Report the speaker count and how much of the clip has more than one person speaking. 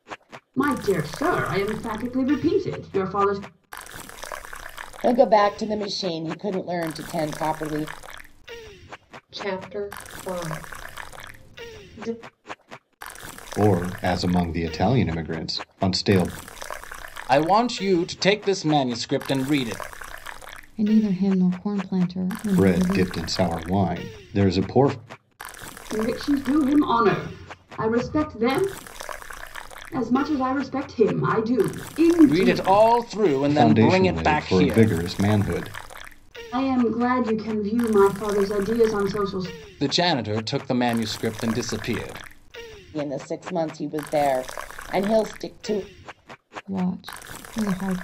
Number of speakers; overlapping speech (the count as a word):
six, about 6%